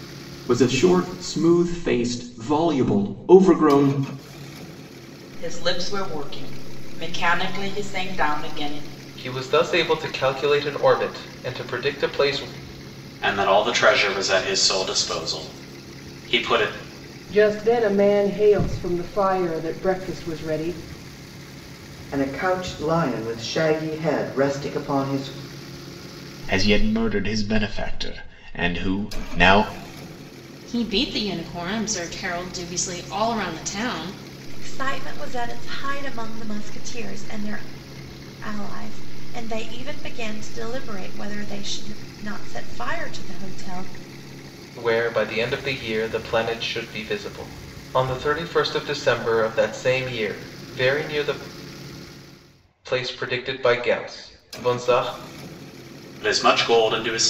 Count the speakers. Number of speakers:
9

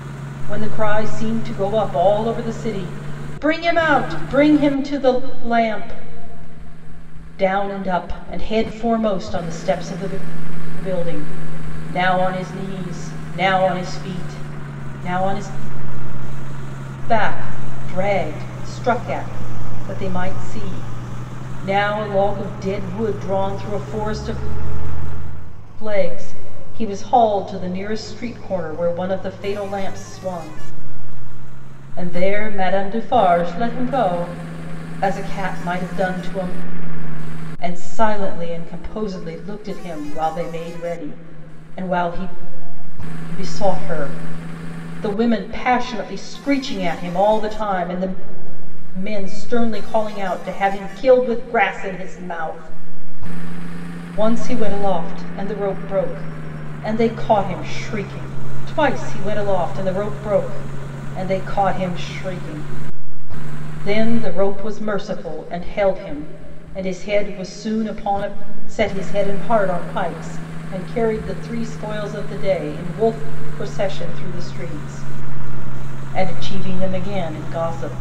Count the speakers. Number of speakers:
1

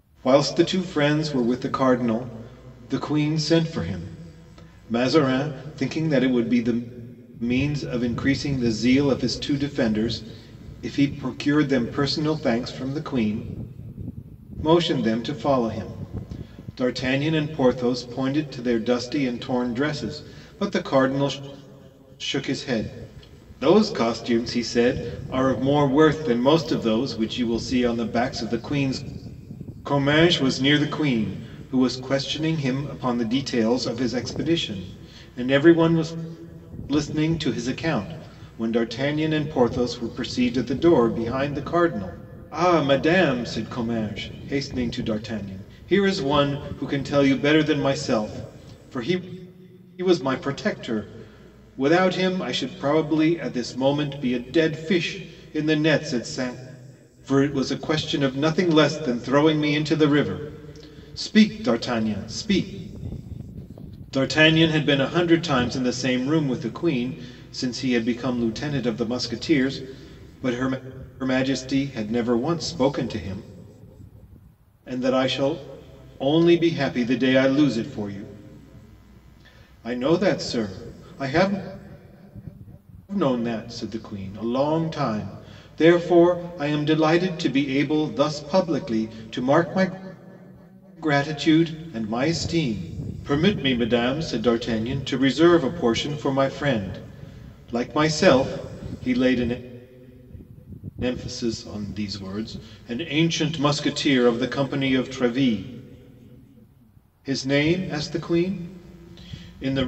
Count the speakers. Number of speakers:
1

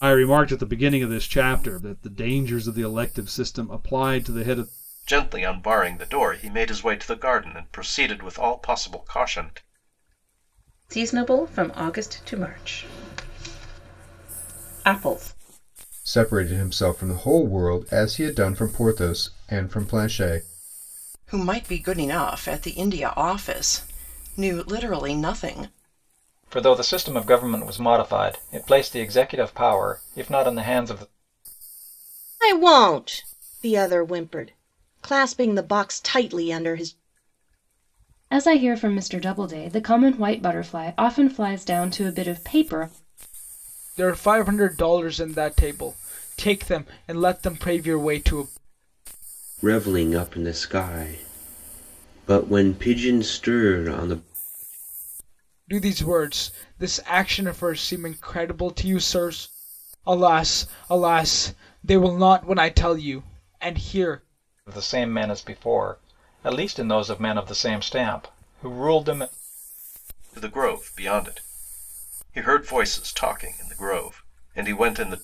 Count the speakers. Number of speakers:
10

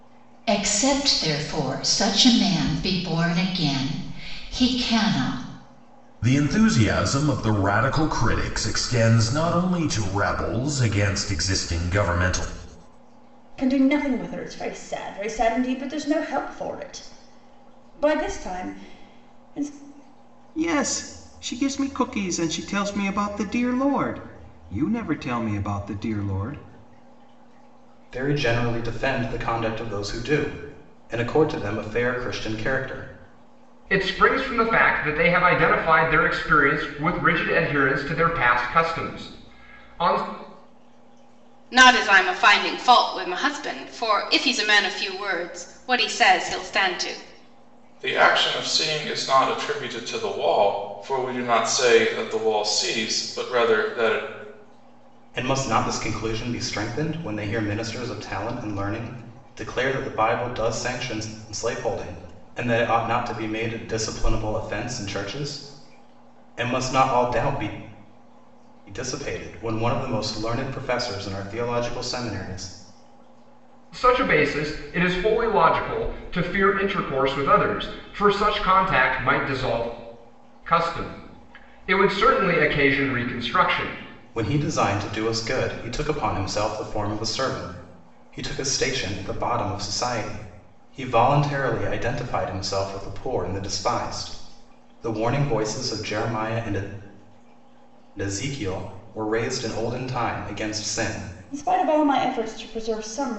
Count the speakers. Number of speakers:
8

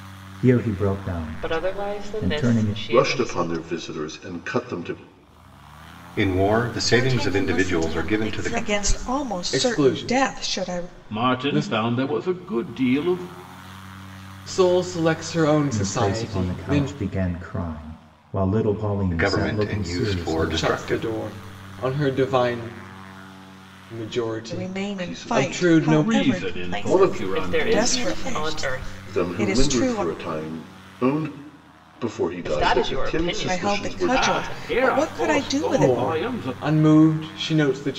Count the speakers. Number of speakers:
8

